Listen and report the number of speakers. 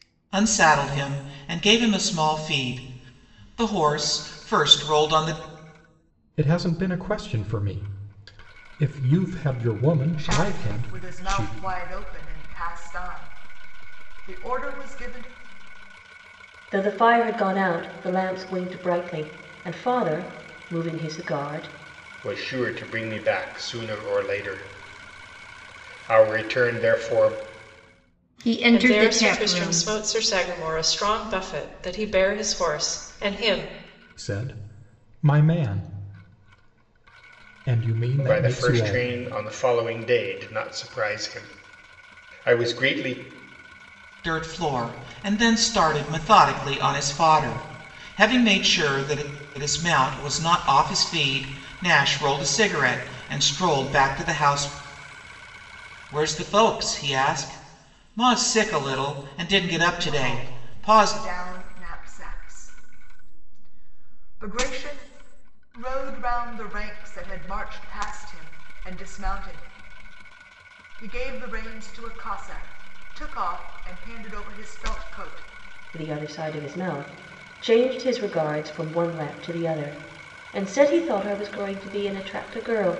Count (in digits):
7